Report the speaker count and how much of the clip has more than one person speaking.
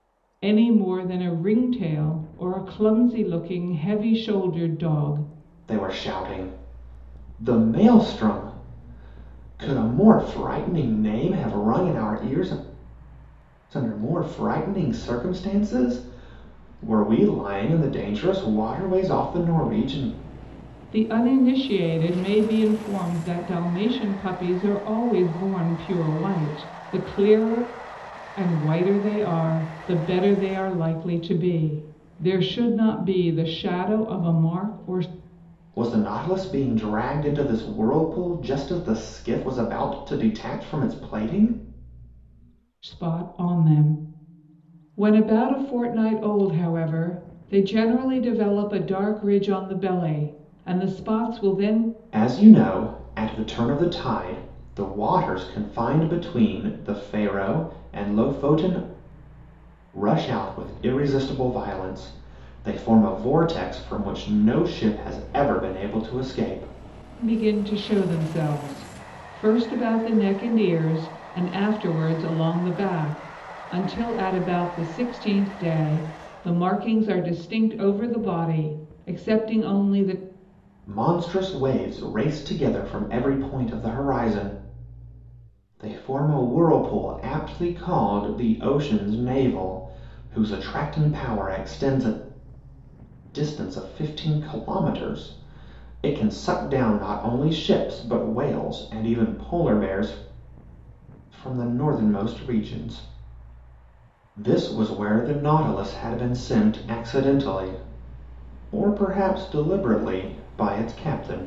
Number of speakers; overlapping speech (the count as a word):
two, no overlap